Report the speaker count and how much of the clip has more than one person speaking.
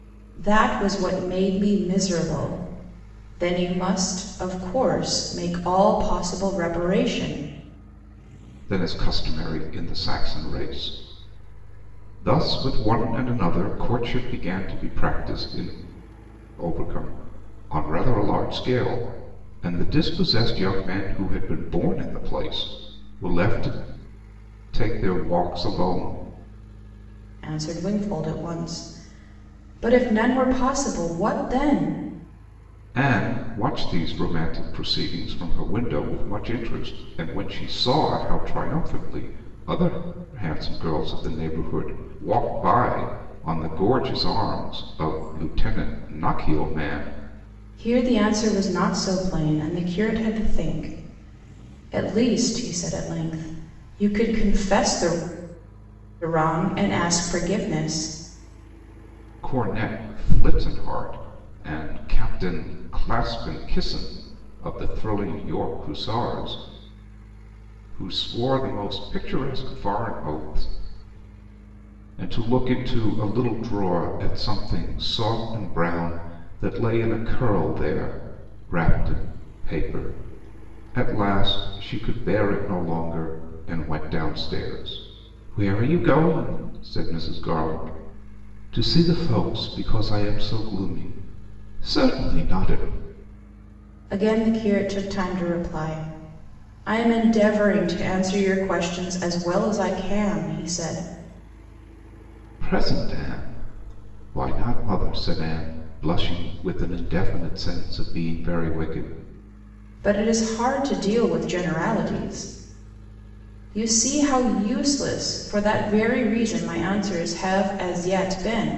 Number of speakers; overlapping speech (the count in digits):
2, no overlap